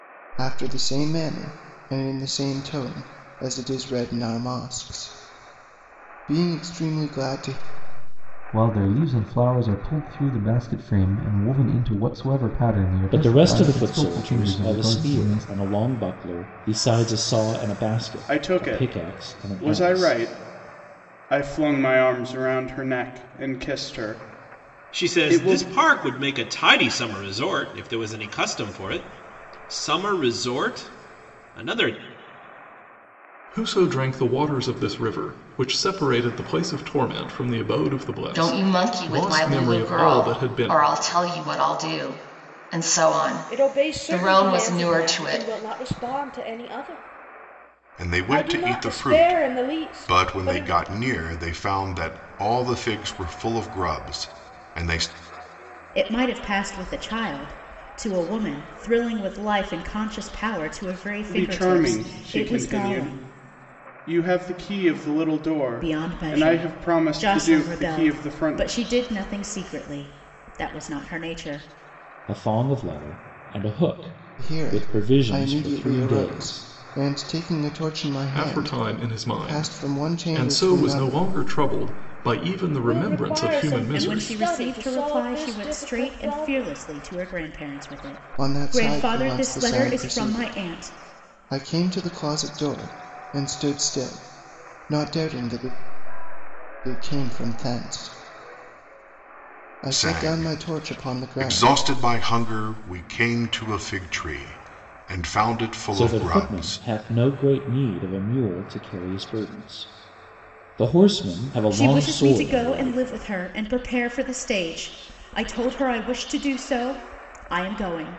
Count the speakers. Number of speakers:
ten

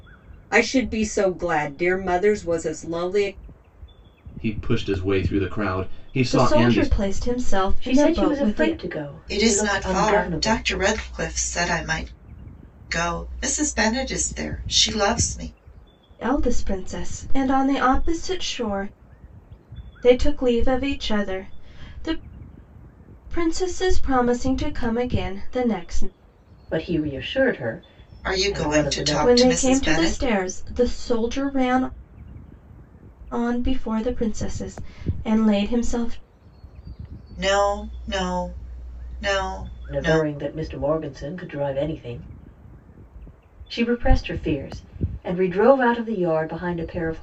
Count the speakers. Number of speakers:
five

